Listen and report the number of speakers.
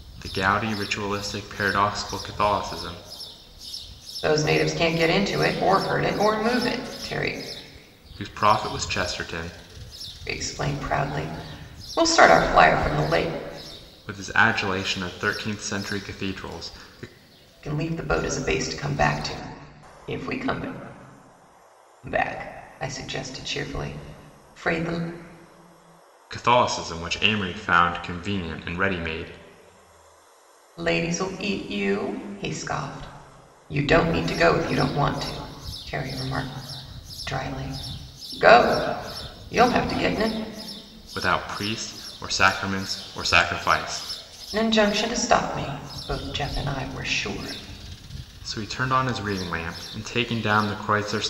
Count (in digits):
2